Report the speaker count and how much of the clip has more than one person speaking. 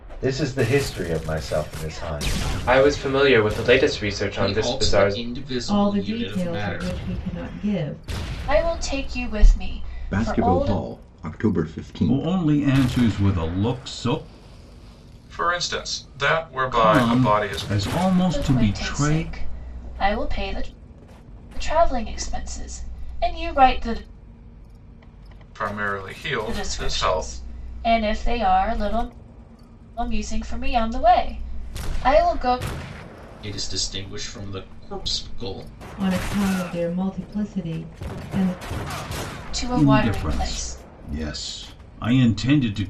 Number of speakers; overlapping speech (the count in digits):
8, about 17%